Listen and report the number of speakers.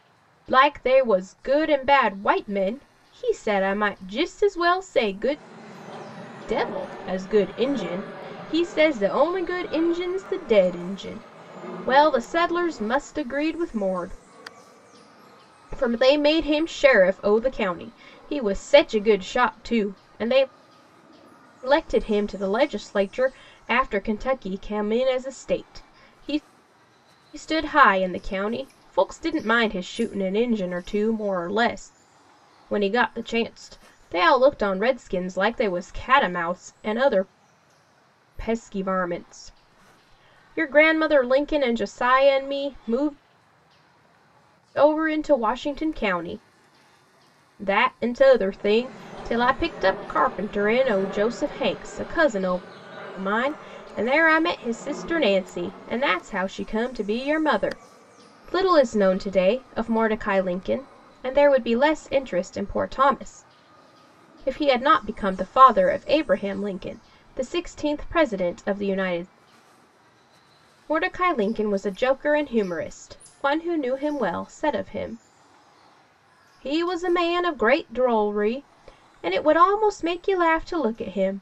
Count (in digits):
1